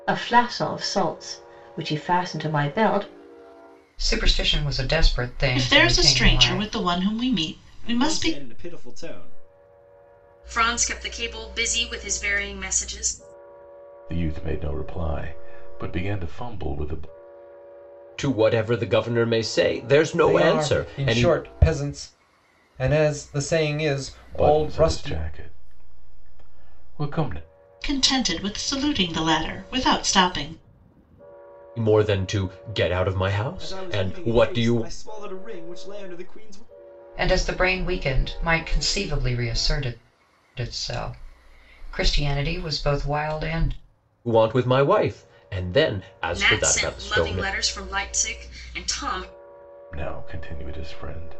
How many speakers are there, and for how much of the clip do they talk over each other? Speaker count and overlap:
8, about 12%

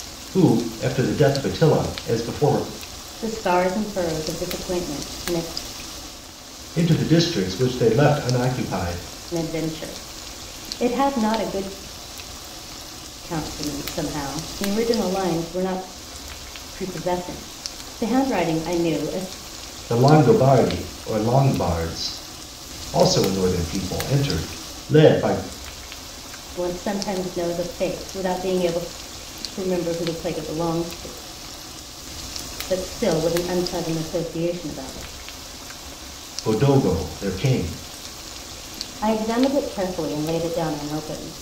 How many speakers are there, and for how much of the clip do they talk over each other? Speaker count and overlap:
2, no overlap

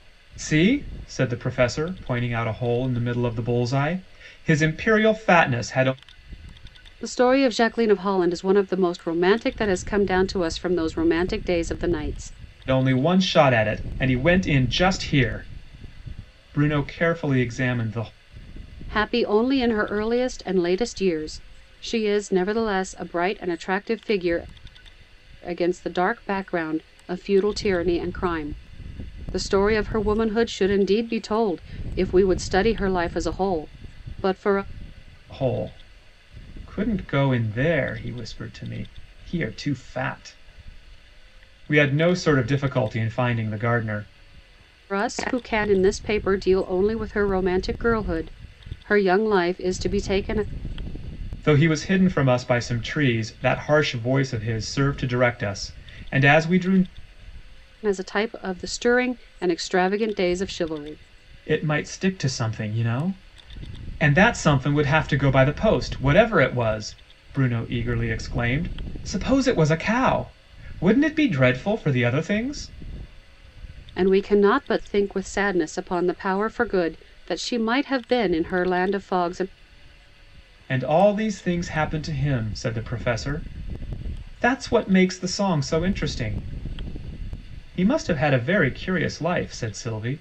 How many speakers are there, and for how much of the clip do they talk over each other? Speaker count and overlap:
2, no overlap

